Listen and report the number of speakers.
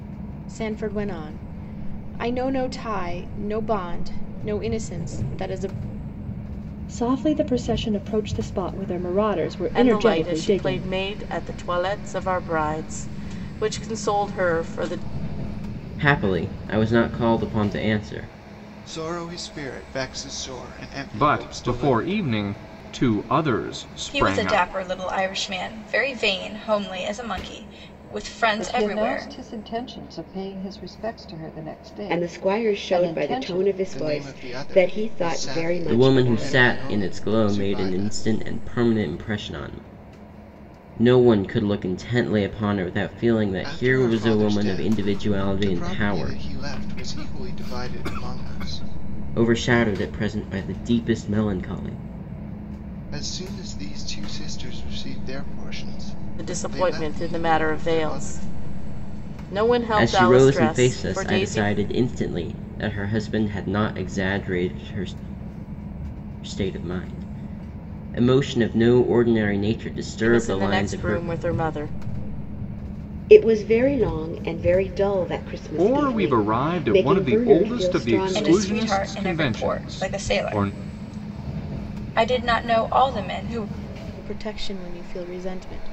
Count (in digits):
9